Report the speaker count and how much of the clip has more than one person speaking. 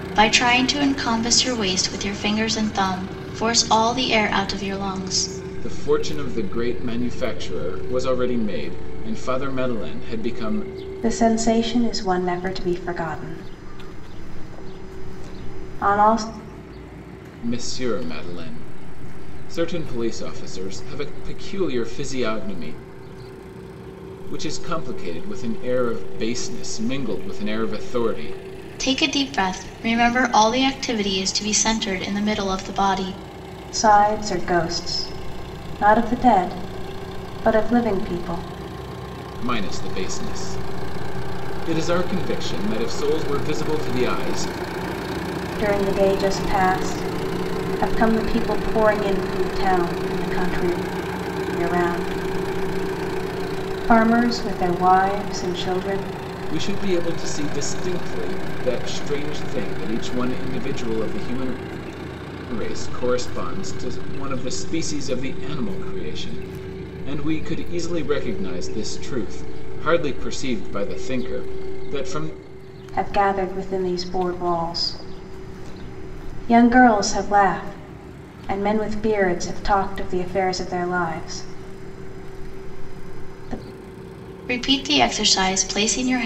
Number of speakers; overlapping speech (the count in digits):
3, no overlap